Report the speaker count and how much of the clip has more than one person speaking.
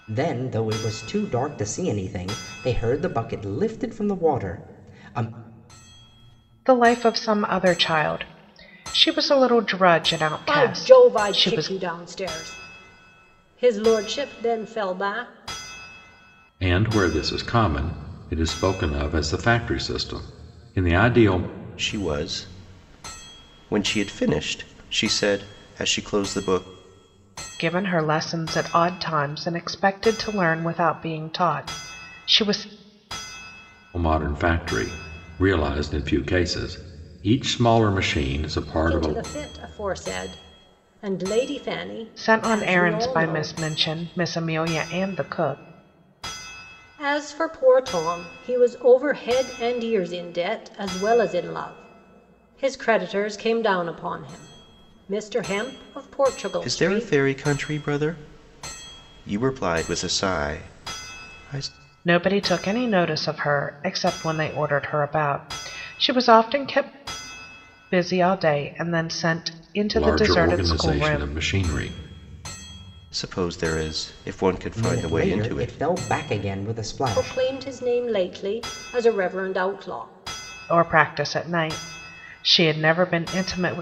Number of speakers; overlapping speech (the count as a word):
five, about 8%